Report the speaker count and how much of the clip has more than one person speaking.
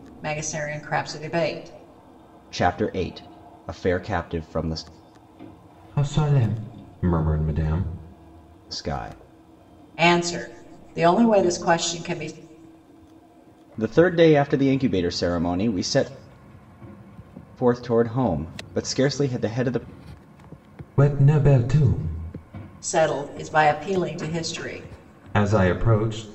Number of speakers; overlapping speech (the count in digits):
3, no overlap